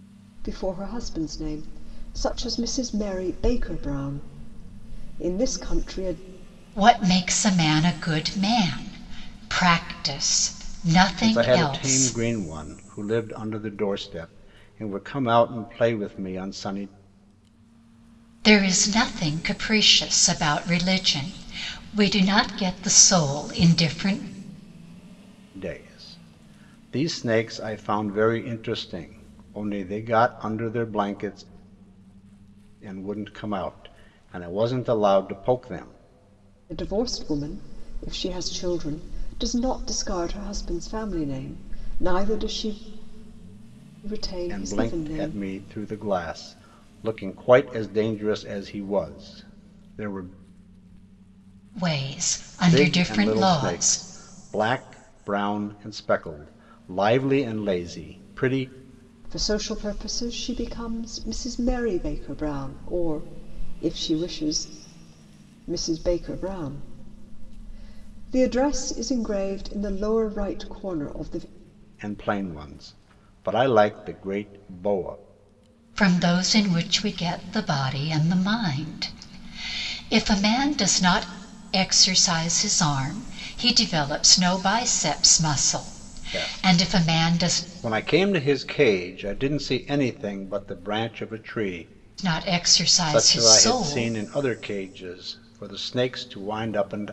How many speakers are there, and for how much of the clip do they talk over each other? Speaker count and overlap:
3, about 6%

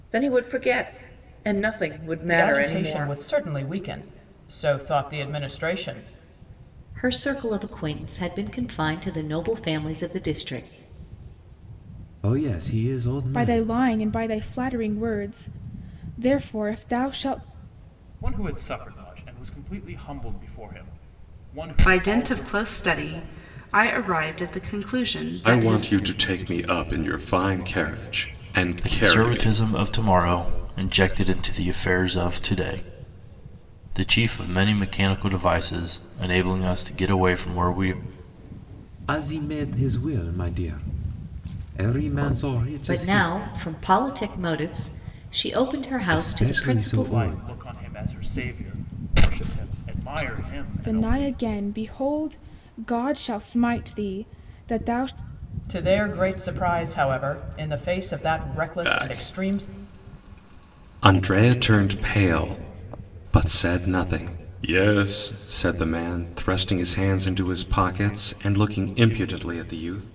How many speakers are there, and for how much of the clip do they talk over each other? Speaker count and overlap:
9, about 10%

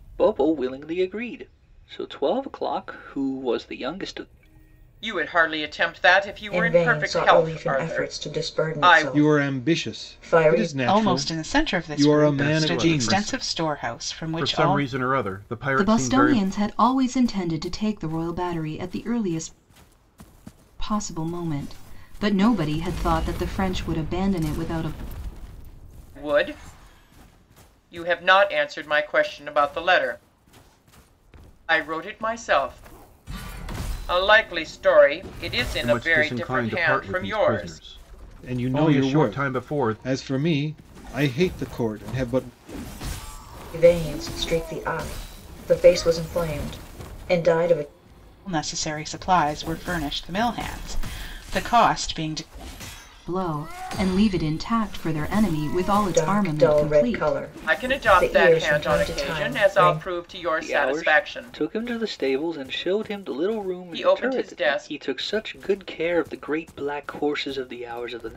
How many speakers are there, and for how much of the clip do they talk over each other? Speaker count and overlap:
7, about 27%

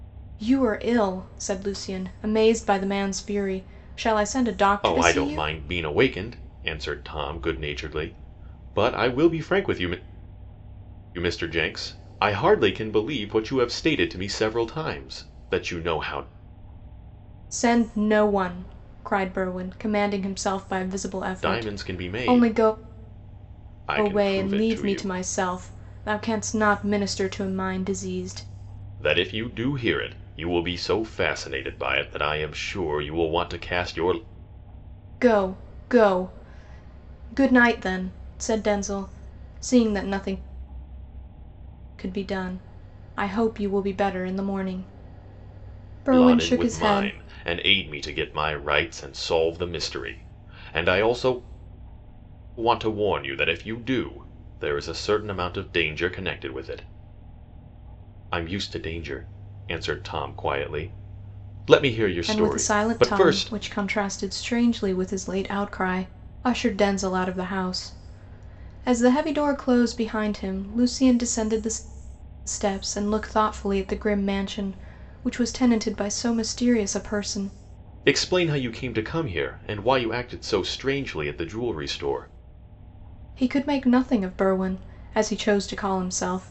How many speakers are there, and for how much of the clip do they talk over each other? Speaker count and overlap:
2, about 6%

